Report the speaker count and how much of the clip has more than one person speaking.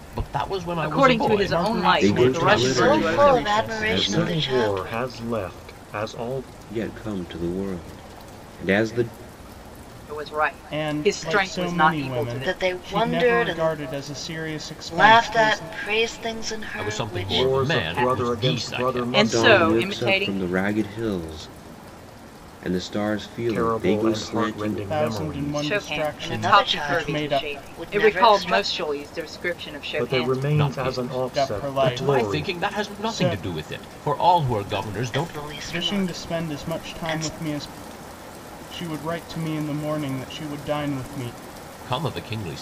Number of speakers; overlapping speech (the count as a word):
six, about 54%